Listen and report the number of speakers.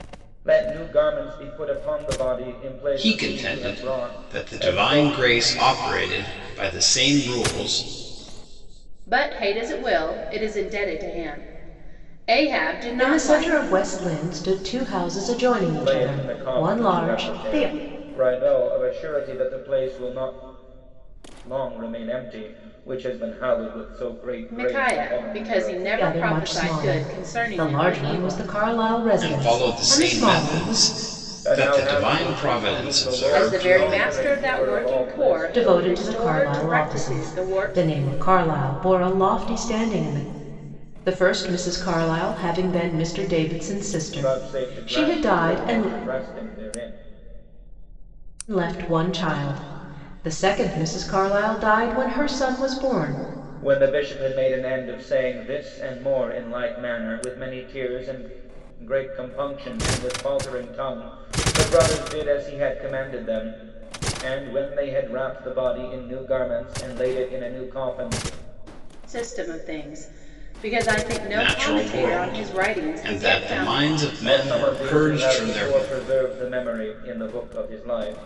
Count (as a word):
four